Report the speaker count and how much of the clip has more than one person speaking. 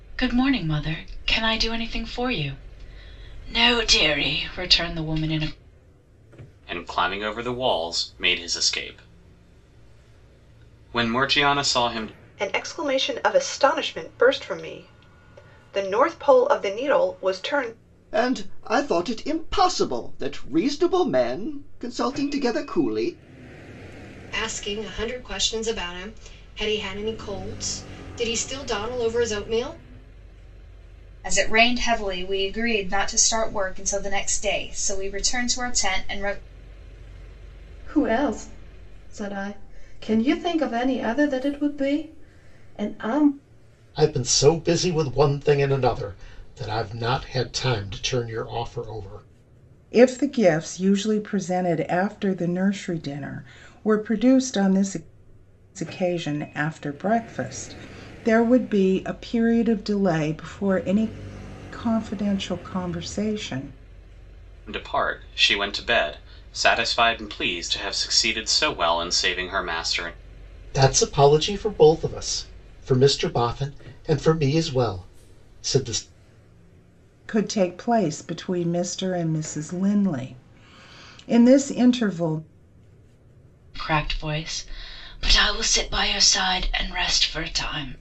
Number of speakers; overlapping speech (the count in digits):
9, no overlap